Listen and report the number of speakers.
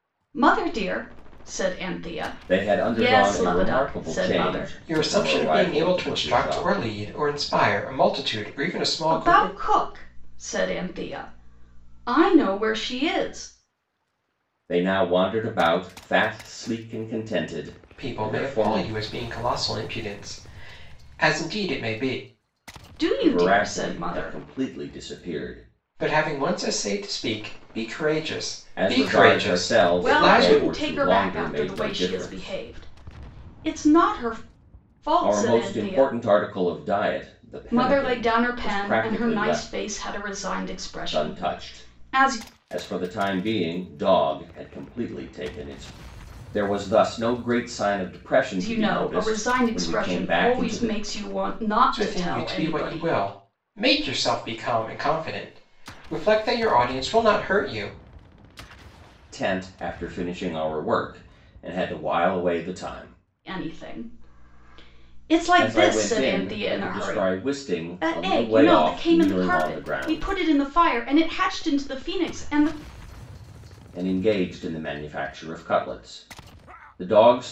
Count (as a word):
three